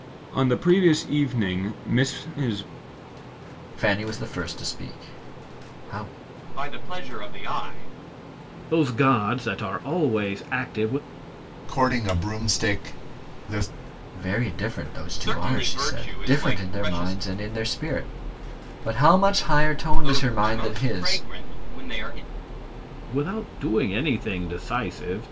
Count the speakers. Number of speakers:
five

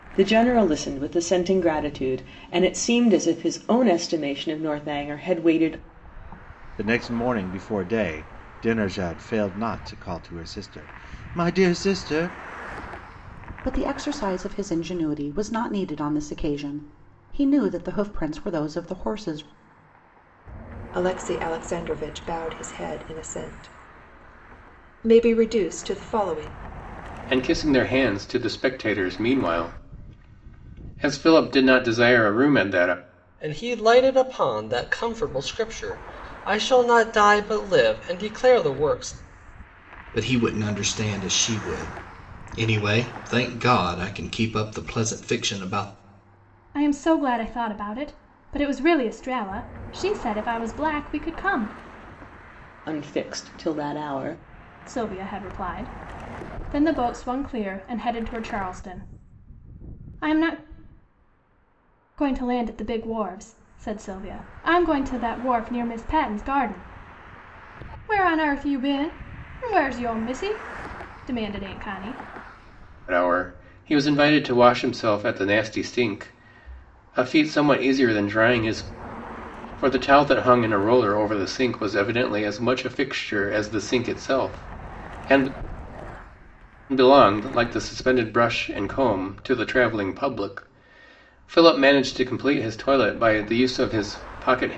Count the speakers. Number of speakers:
eight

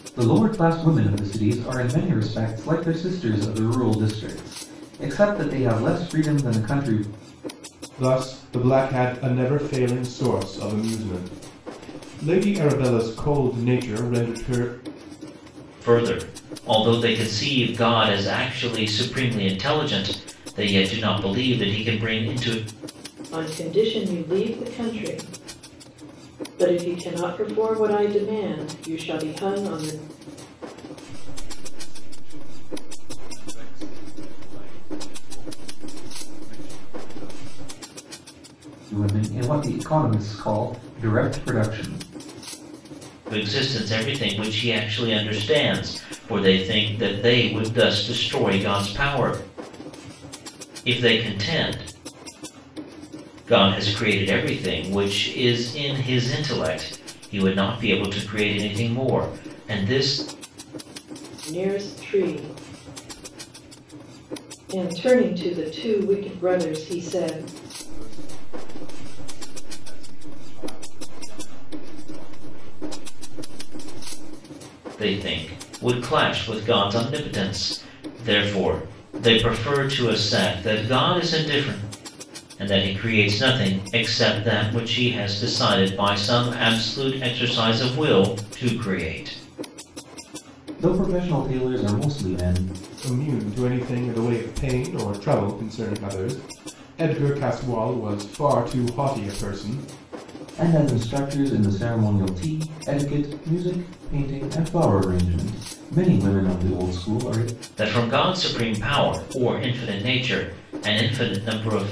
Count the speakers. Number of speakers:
five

